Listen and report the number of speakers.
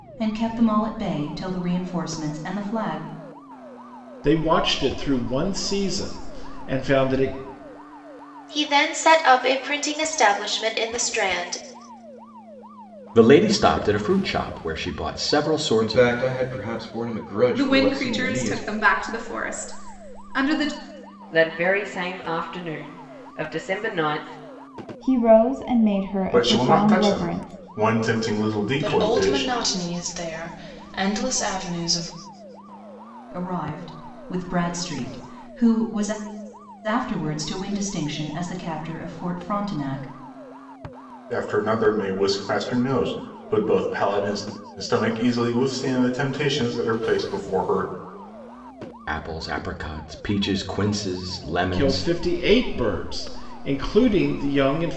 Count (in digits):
10